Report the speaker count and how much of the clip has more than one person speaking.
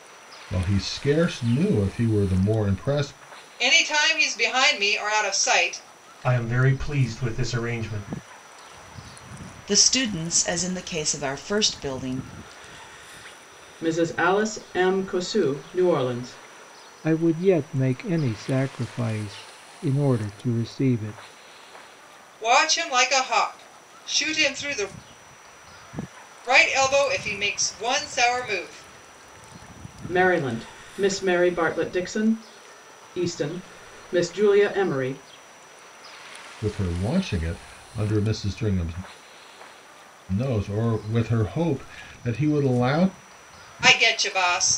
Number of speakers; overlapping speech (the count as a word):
six, no overlap